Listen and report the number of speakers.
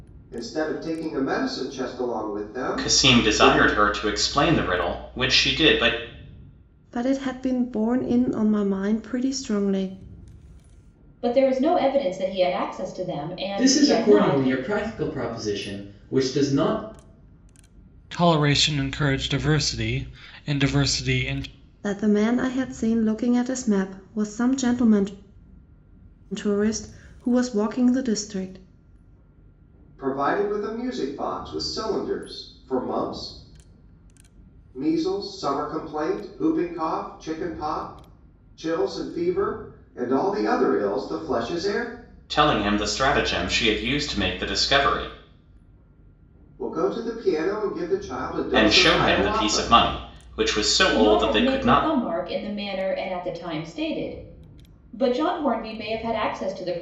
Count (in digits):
6